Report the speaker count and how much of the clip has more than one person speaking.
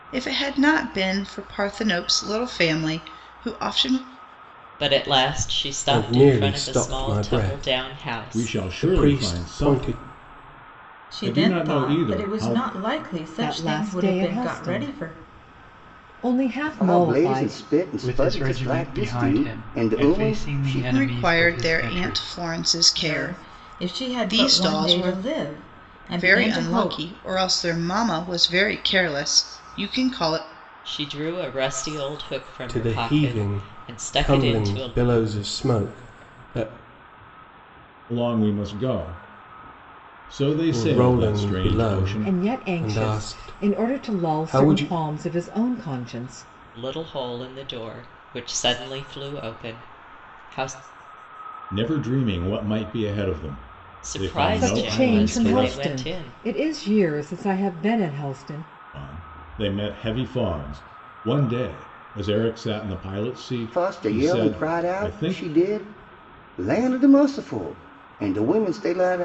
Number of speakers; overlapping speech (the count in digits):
8, about 39%